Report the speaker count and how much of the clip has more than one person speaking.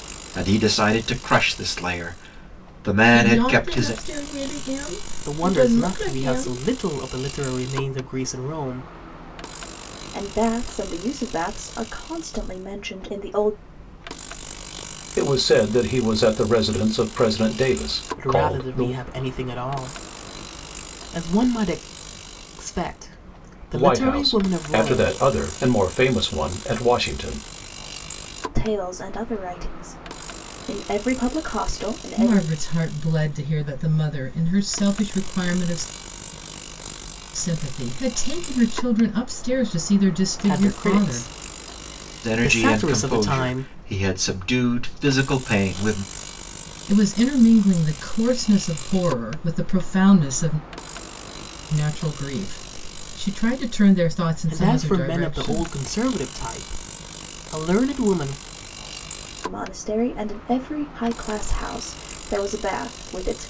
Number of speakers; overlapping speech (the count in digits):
5, about 13%